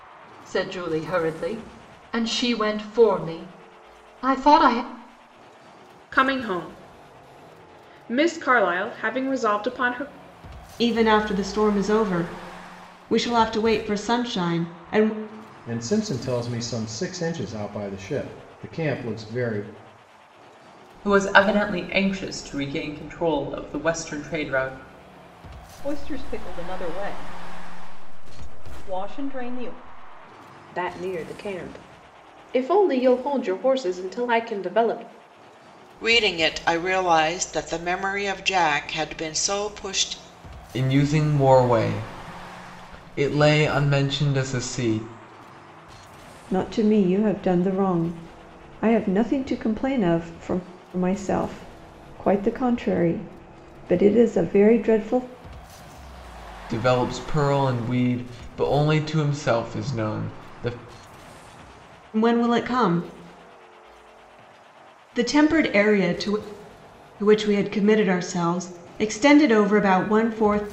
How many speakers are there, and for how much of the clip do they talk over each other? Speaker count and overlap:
ten, no overlap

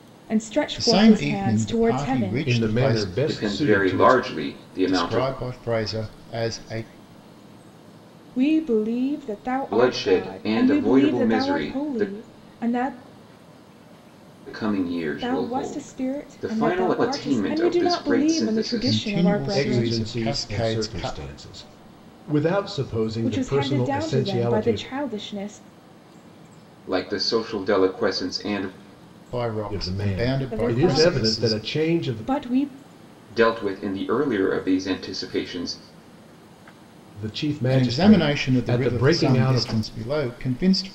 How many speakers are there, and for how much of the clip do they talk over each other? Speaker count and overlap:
four, about 46%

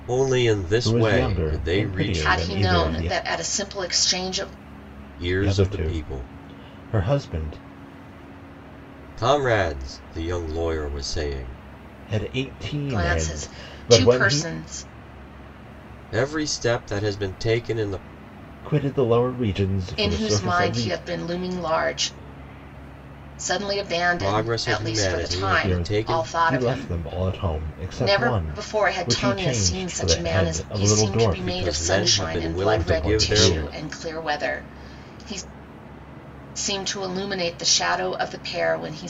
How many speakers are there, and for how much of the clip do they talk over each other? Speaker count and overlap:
three, about 40%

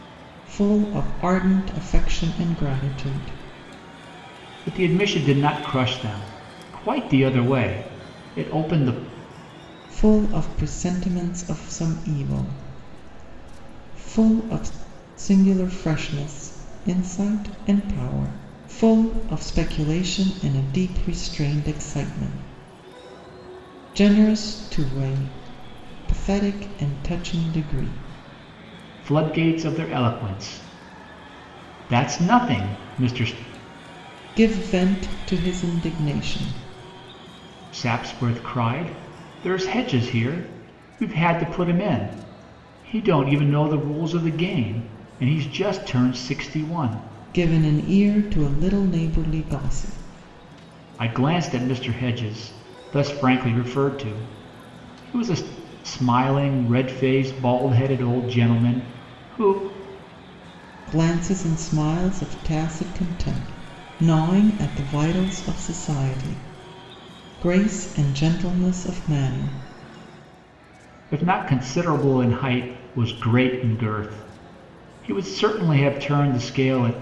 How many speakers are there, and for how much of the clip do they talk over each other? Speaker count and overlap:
two, no overlap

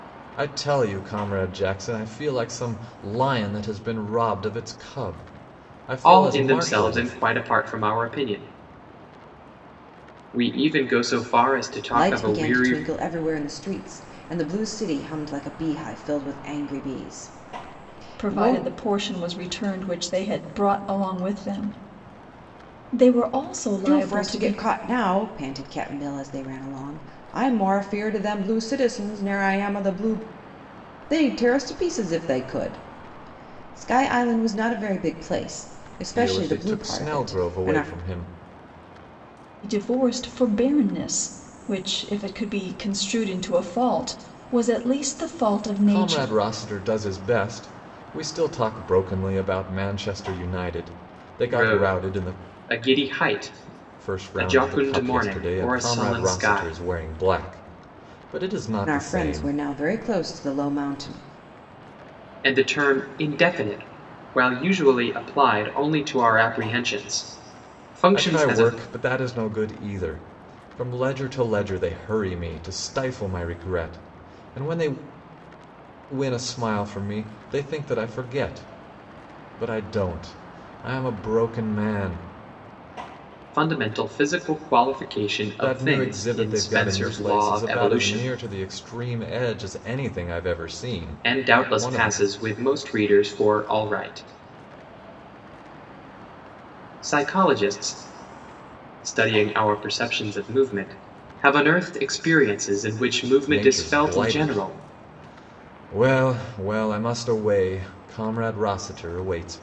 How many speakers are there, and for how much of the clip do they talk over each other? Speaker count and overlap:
four, about 14%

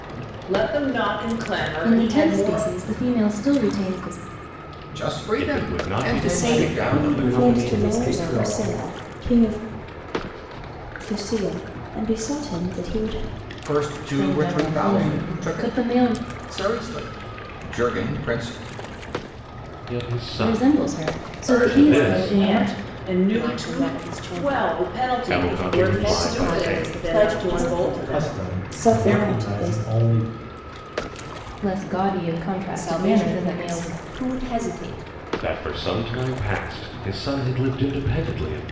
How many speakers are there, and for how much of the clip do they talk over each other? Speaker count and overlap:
seven, about 41%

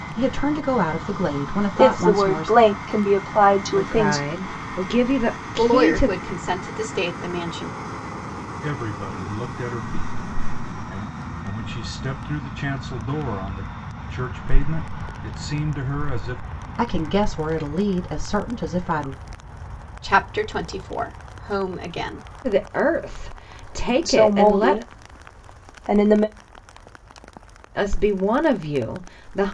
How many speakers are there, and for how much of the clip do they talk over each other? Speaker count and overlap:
five, about 9%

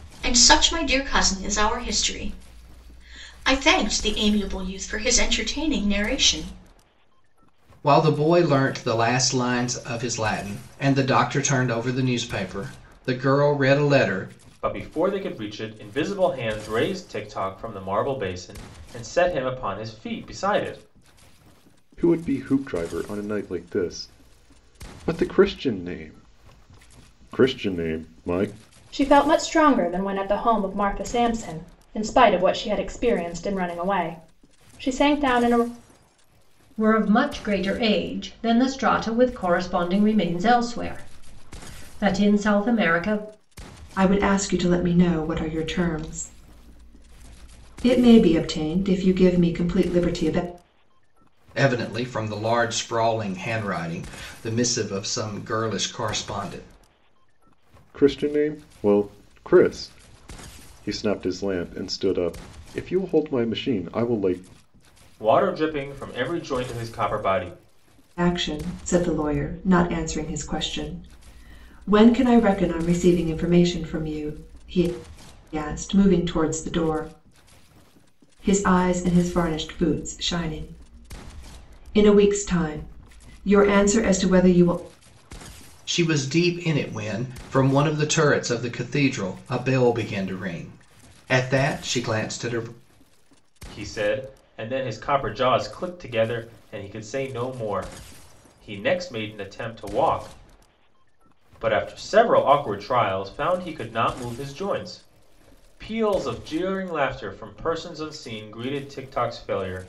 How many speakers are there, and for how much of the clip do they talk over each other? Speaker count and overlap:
seven, no overlap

